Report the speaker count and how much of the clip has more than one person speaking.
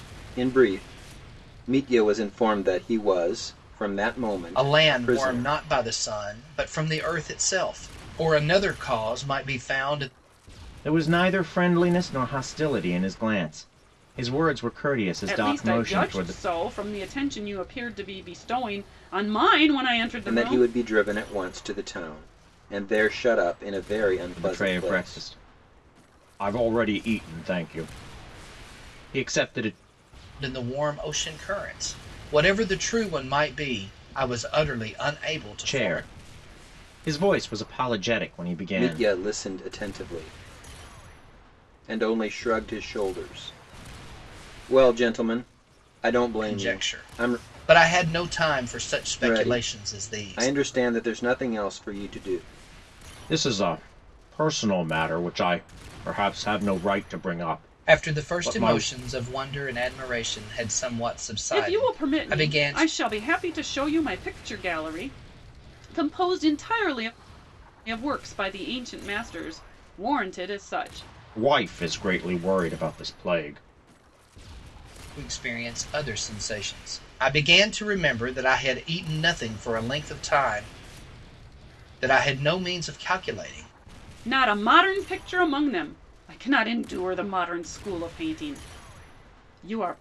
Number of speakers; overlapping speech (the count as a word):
four, about 10%